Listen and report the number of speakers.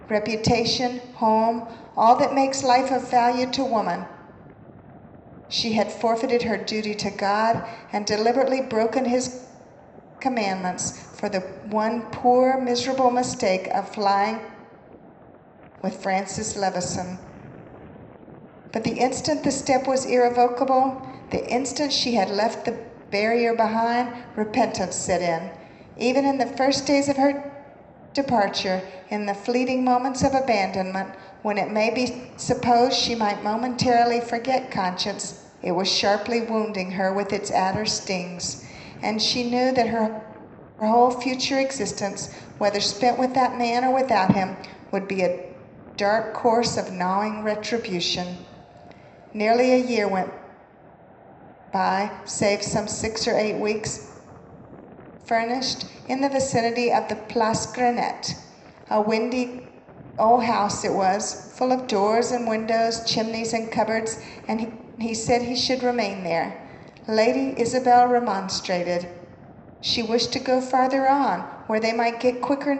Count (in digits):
1